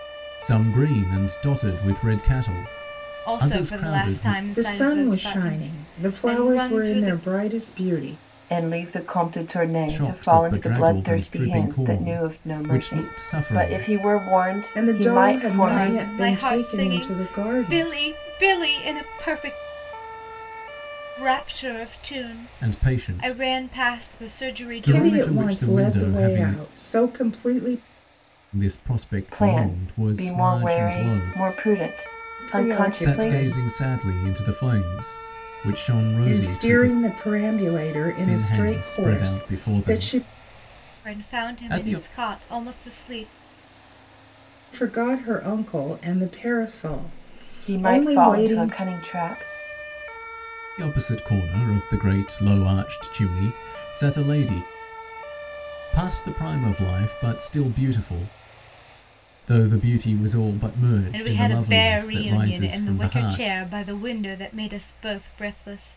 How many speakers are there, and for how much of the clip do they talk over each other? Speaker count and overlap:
four, about 39%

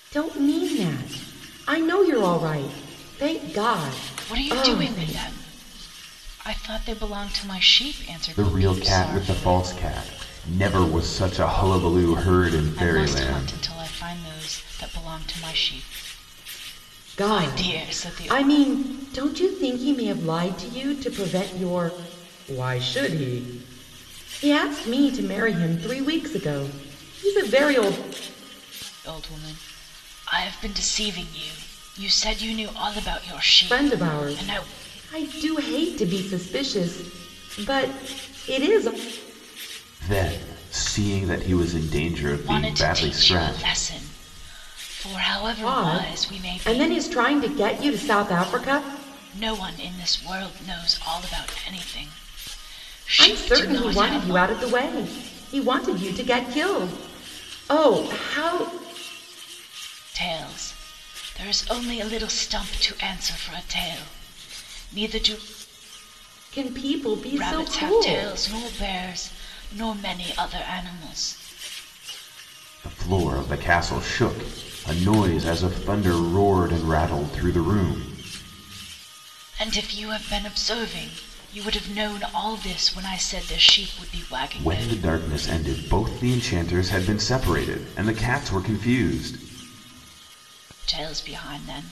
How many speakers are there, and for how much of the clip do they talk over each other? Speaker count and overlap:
three, about 12%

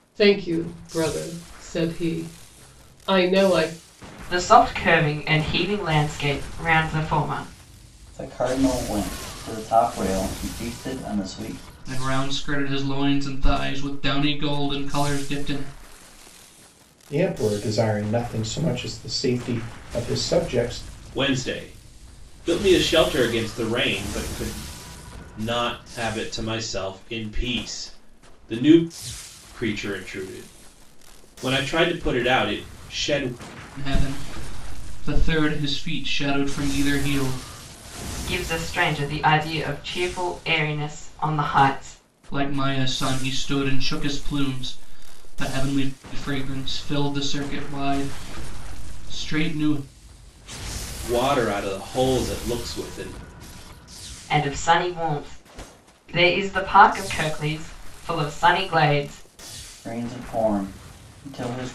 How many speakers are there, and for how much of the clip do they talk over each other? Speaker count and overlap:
six, no overlap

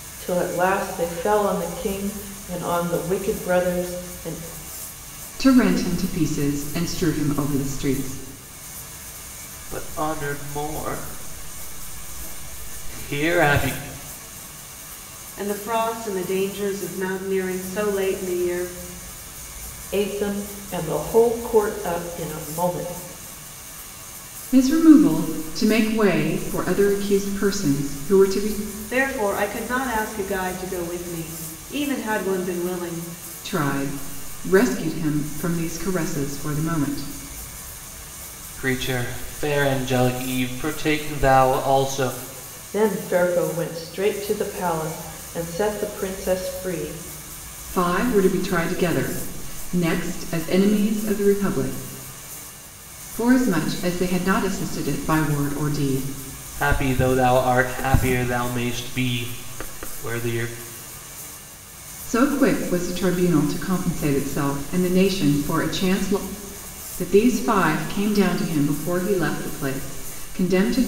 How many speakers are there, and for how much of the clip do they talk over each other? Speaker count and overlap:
four, no overlap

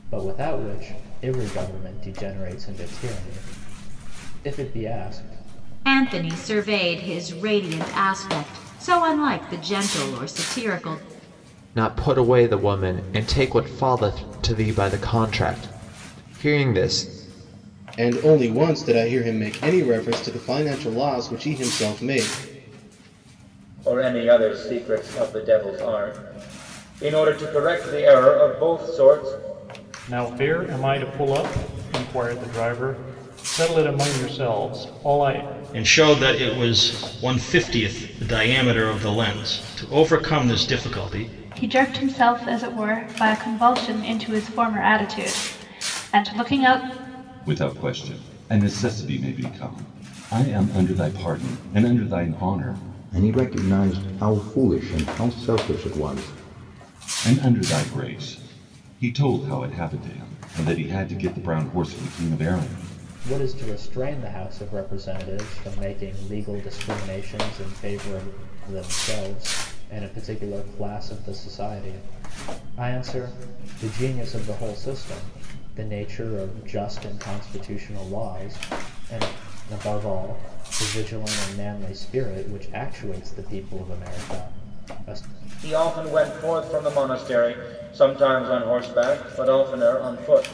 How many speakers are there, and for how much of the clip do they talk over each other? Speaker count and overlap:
ten, no overlap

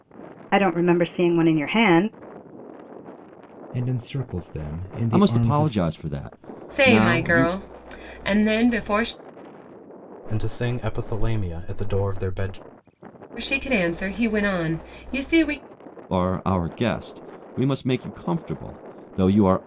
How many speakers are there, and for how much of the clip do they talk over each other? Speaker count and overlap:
five, about 8%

